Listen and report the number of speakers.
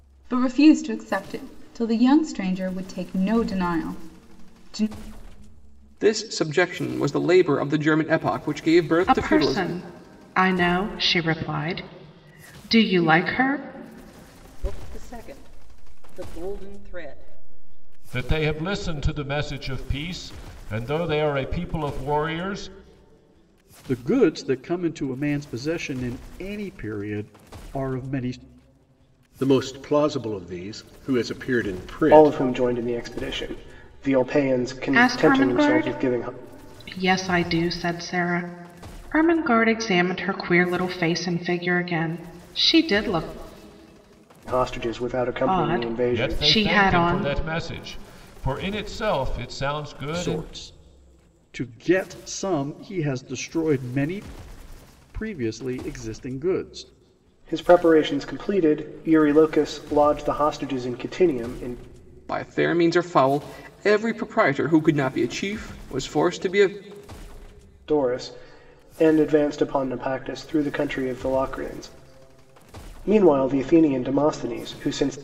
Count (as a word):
eight